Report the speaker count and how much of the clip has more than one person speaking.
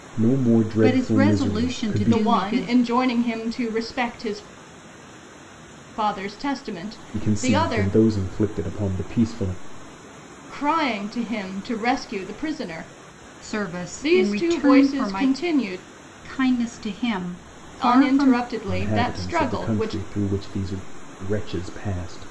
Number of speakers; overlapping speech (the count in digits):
3, about 27%